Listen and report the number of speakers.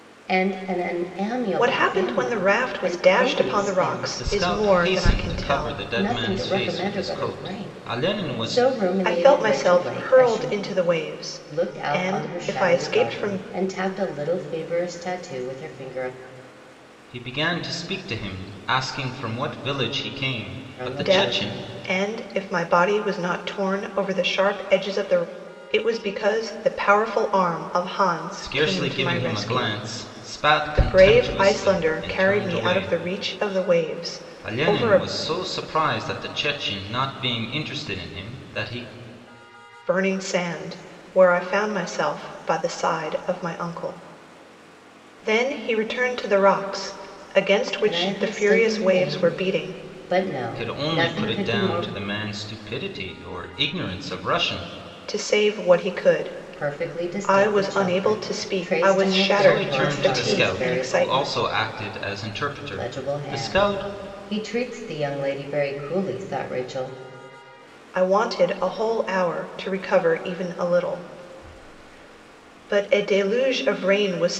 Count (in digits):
3